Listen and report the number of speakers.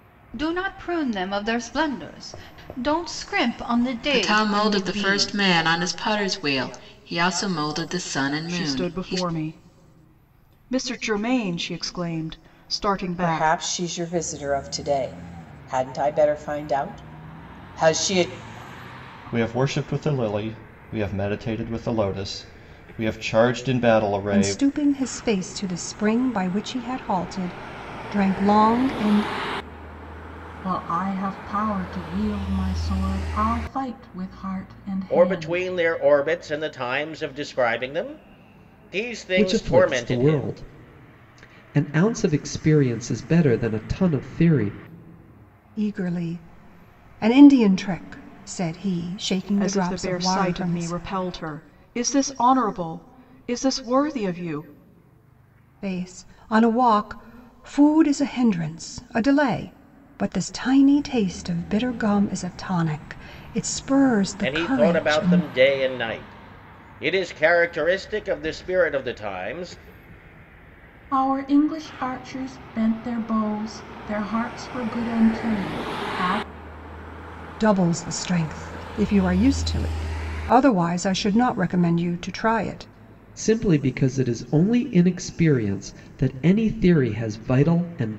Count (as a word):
nine